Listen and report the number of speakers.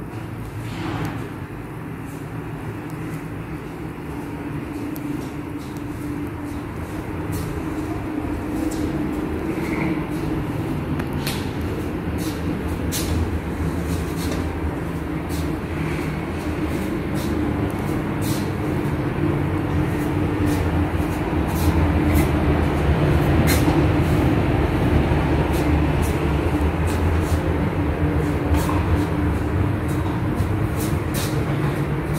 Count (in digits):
0